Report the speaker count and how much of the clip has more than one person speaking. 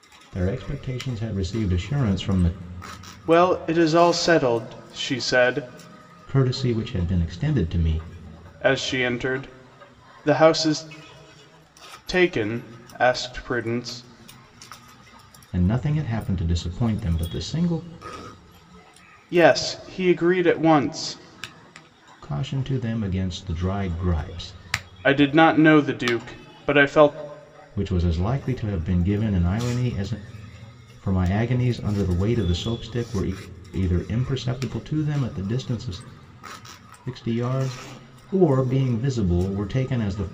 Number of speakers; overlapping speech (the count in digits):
2, no overlap